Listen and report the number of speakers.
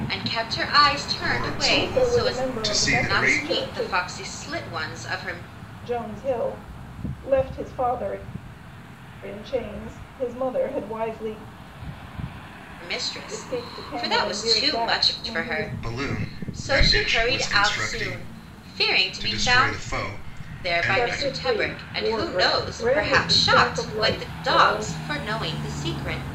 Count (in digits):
3